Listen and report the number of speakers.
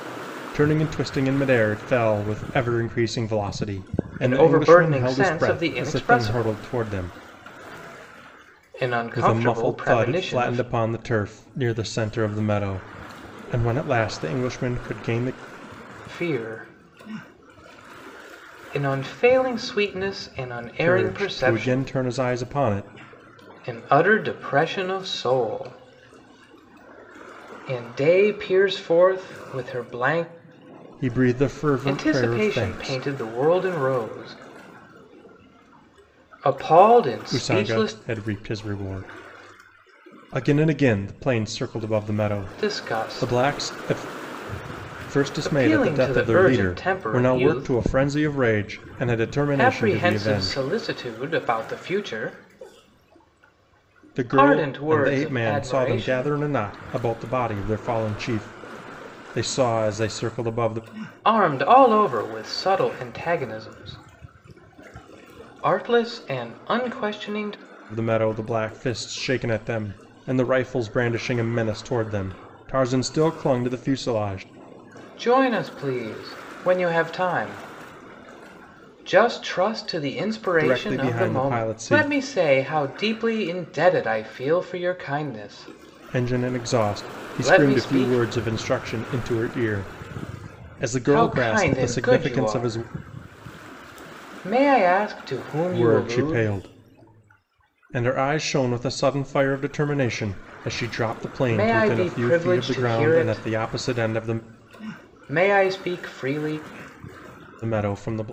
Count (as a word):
two